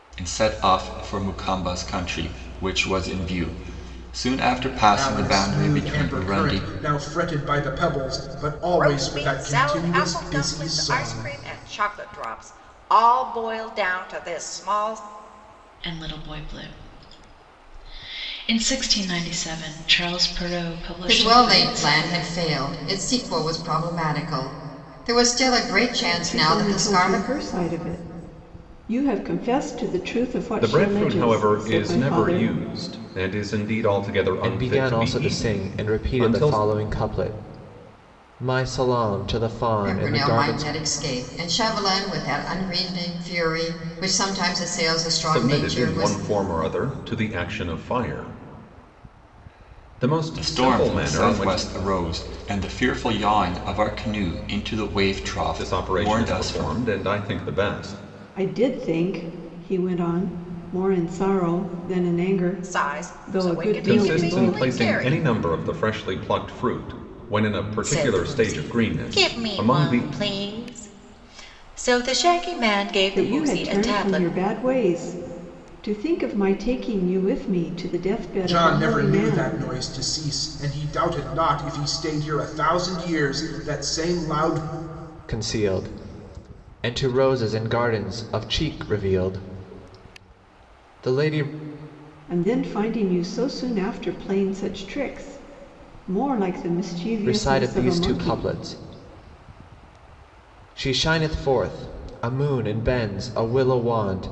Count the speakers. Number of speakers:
eight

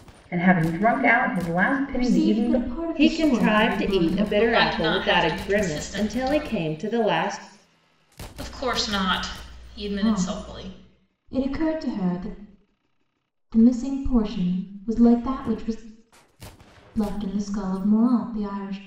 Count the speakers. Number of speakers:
four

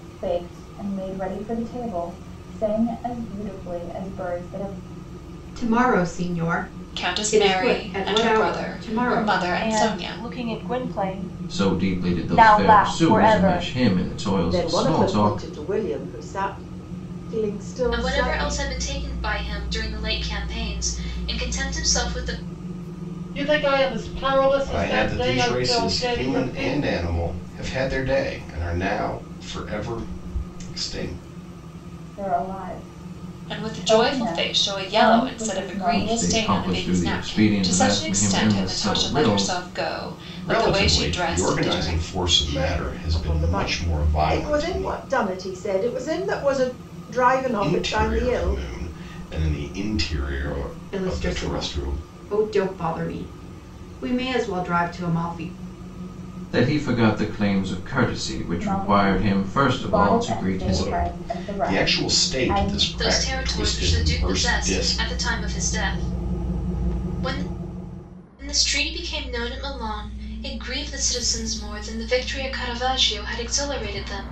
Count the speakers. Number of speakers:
nine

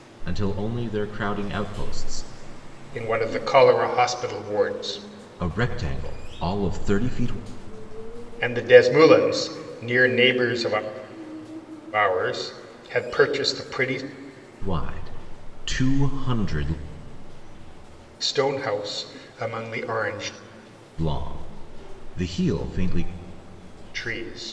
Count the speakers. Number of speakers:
two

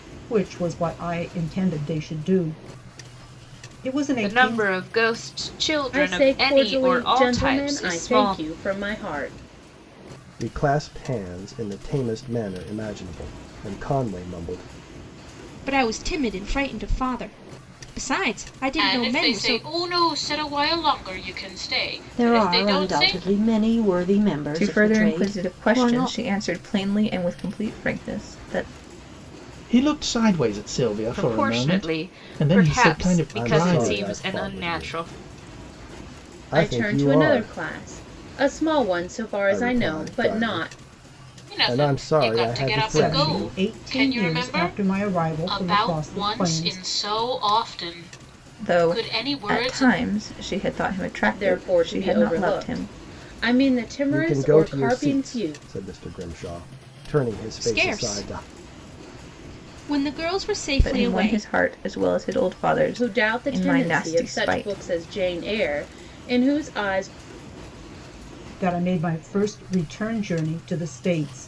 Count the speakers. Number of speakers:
nine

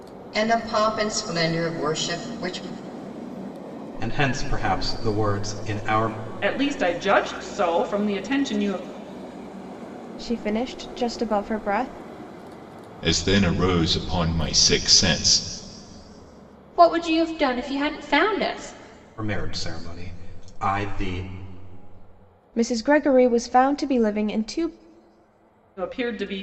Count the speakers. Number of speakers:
six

